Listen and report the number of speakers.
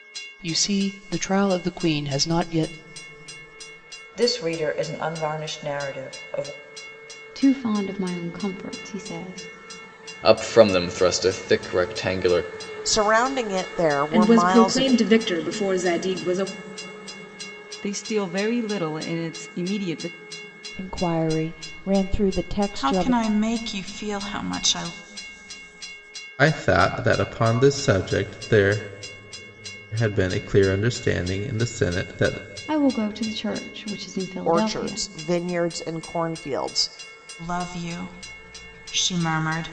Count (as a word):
ten